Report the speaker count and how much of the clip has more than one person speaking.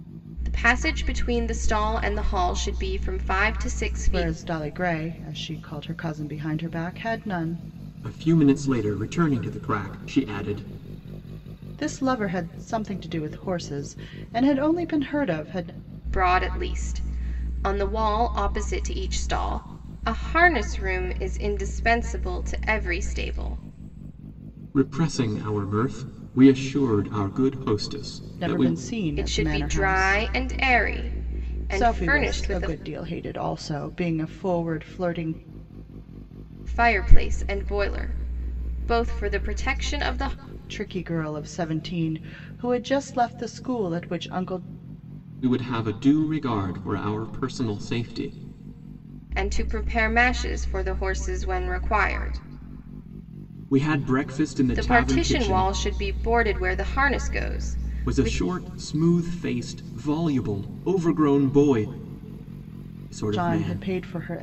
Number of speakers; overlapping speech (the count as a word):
three, about 8%